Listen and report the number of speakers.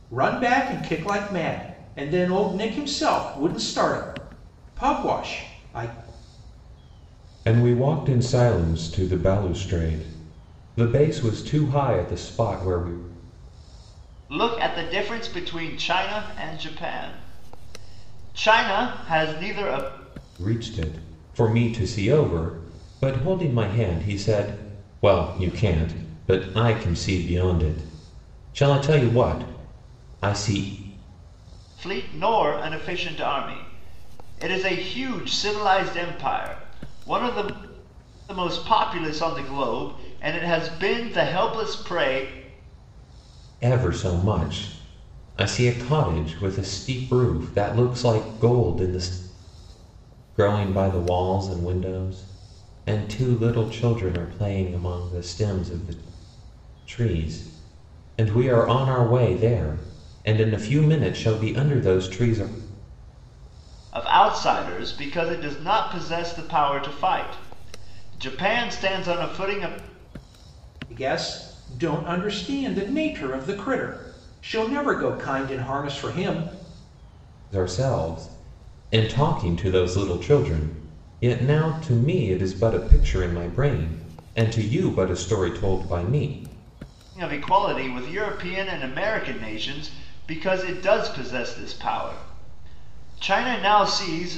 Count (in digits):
3